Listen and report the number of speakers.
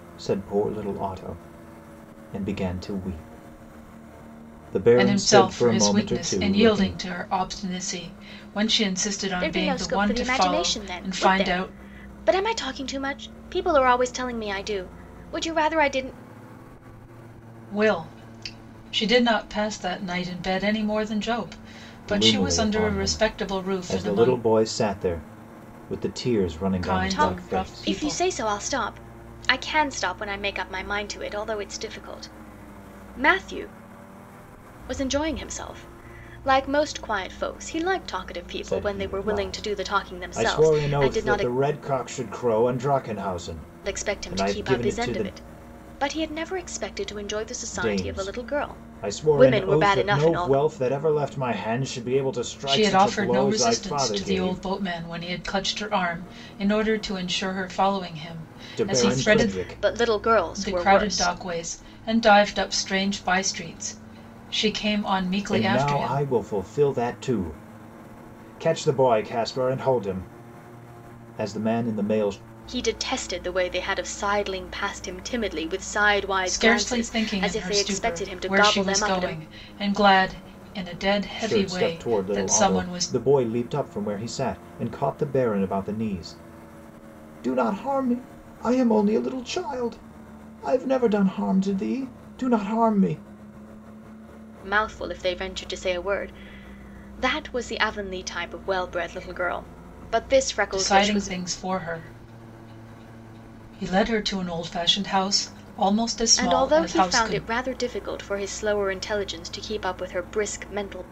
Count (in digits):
3